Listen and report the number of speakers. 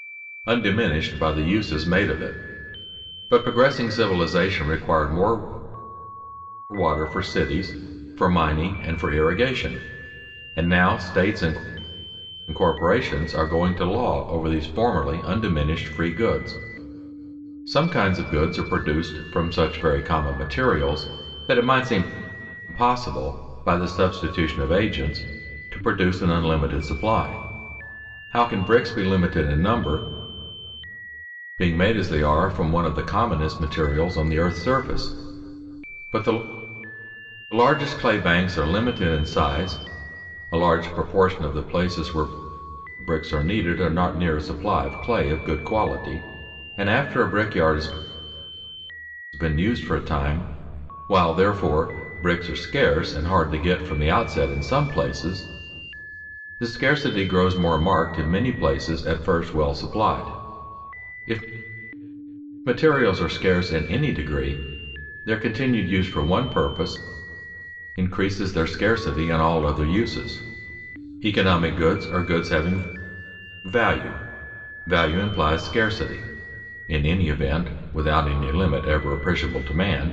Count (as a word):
one